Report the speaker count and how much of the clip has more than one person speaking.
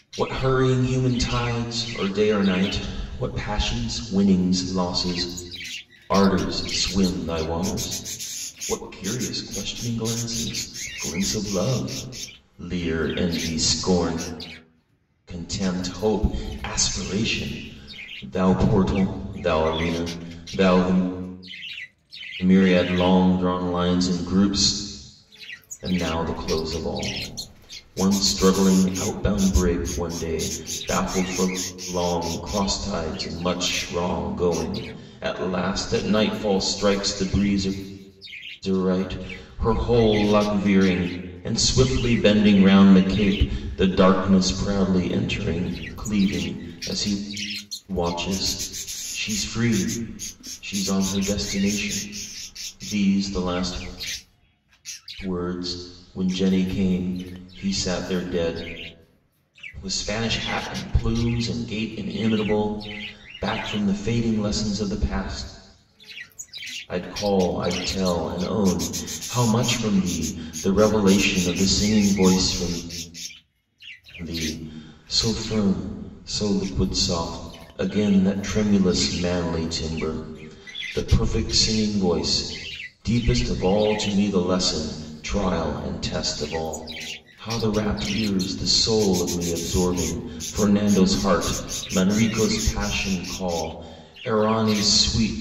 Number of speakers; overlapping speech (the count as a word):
one, no overlap